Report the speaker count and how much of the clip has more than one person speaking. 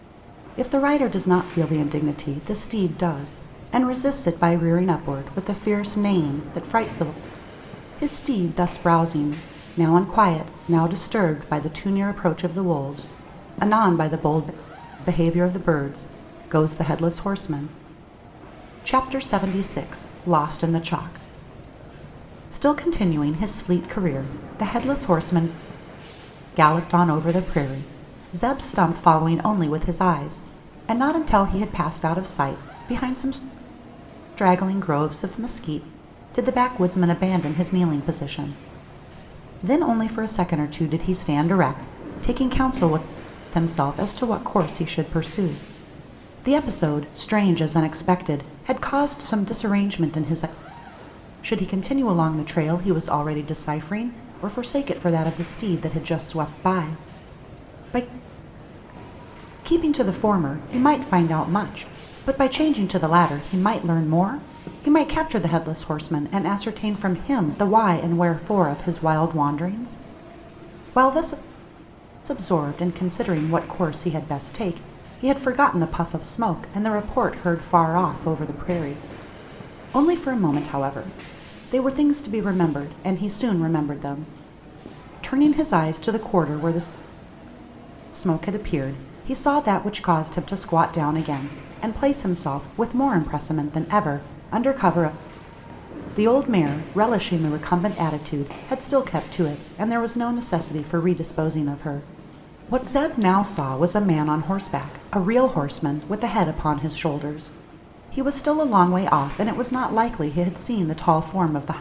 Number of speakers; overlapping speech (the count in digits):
1, no overlap